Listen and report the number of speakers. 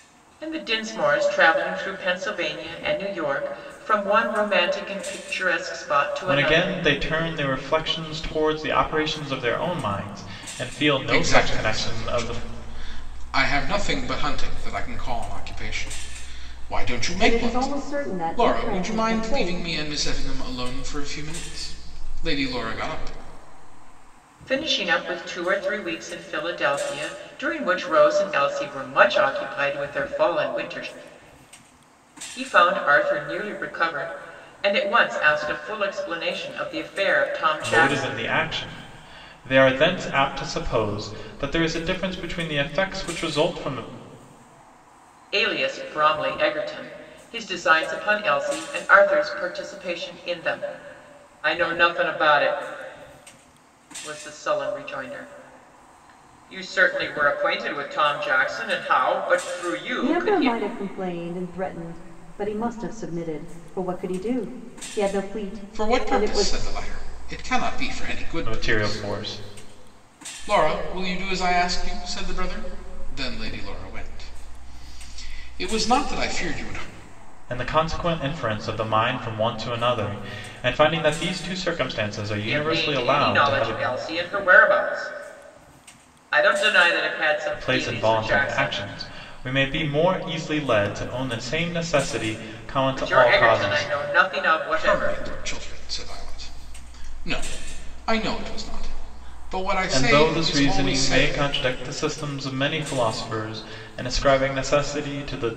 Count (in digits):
4